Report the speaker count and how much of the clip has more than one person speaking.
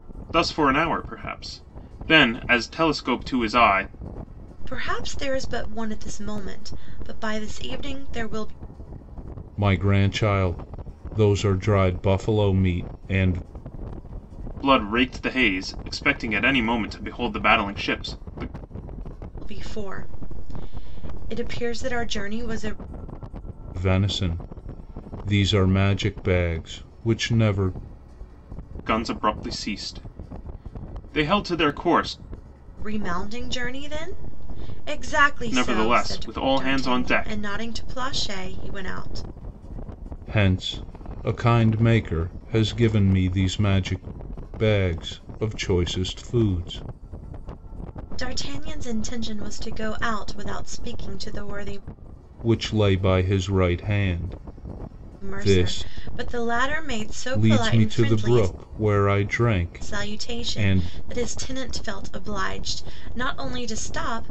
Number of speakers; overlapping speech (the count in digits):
3, about 7%